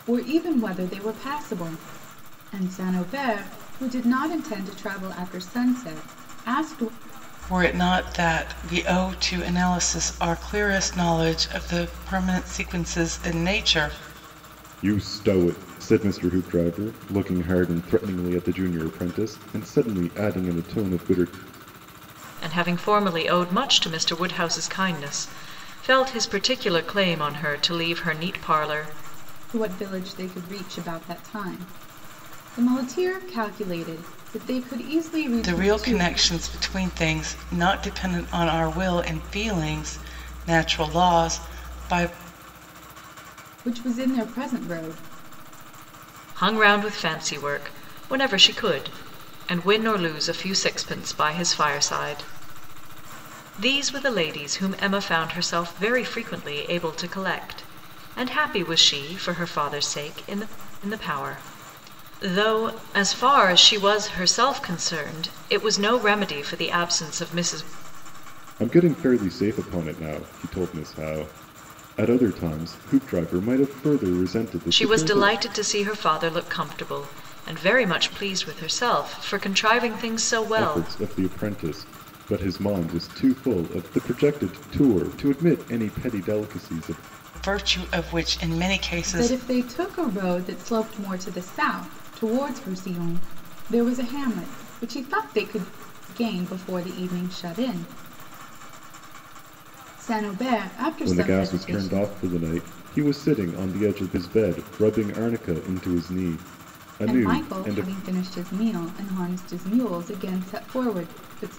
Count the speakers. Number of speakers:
4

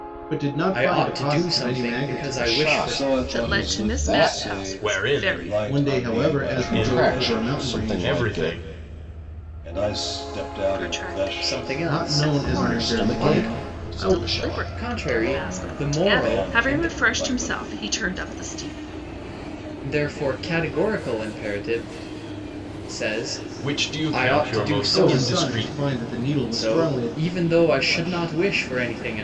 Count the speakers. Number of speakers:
6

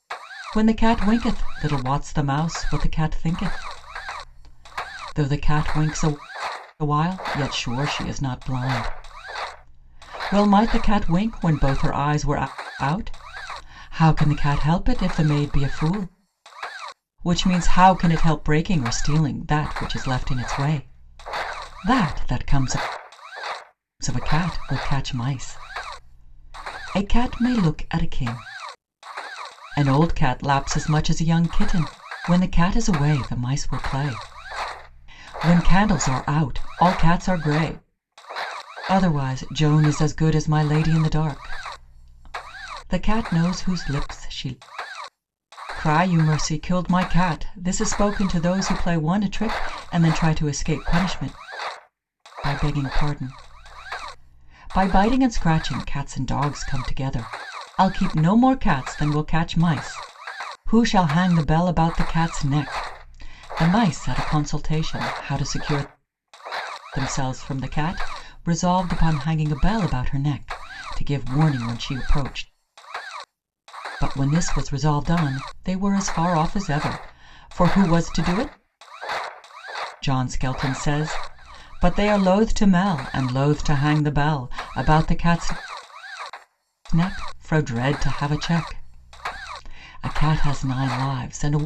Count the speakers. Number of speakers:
1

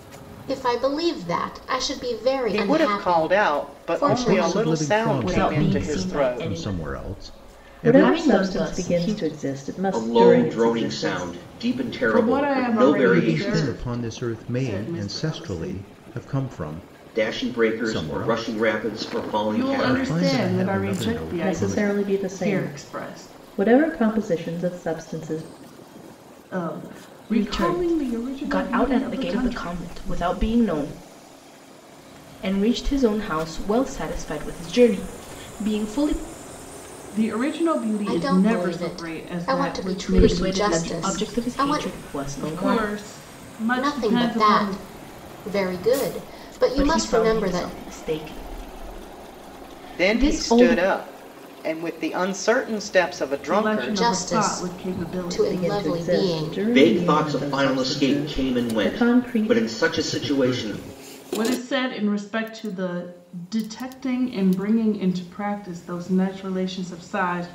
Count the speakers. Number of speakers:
7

